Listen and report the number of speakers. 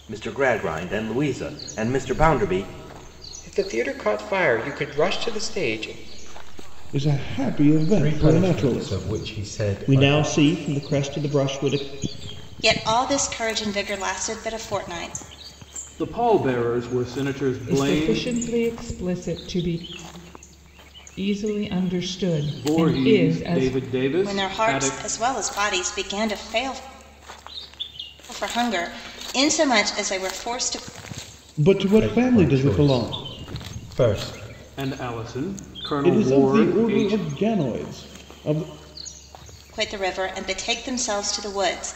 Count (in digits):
9